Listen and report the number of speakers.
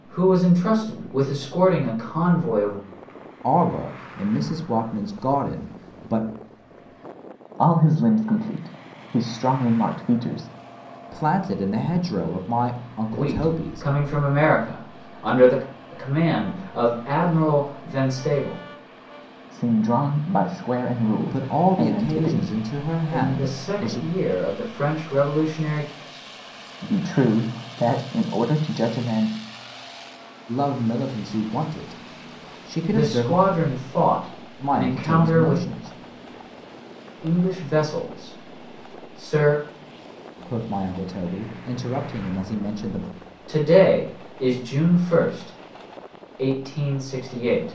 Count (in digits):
3